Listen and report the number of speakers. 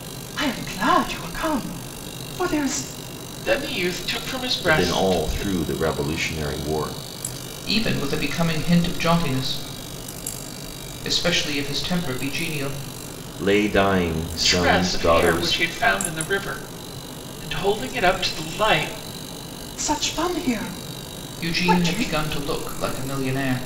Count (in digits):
4